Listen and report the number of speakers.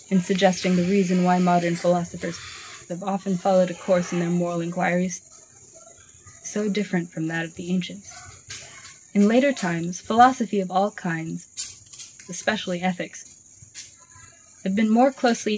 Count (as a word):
one